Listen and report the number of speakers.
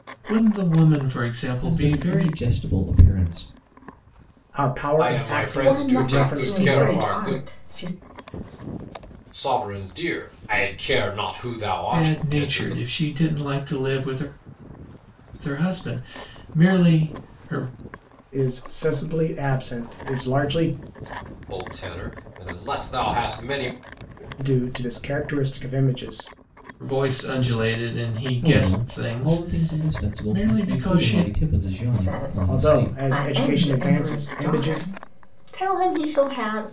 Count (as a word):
five